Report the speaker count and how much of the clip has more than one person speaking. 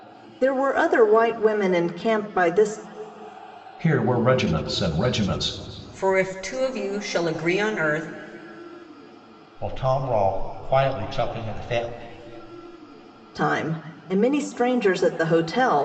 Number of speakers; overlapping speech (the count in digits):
4, no overlap